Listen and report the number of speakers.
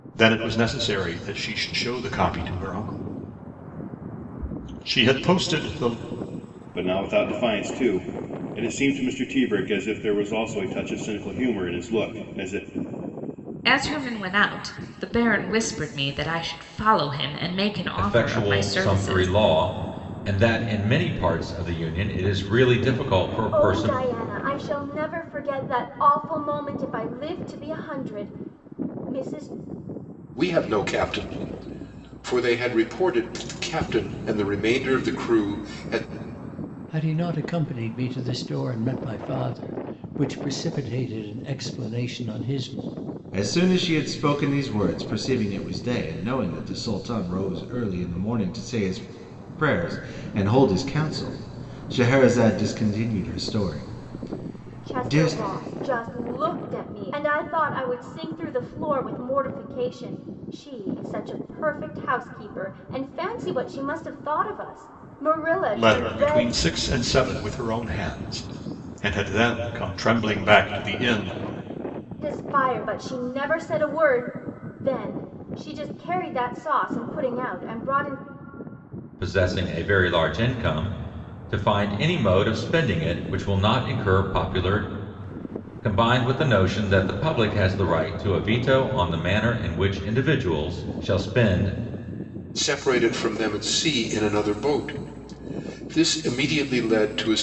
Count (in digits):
8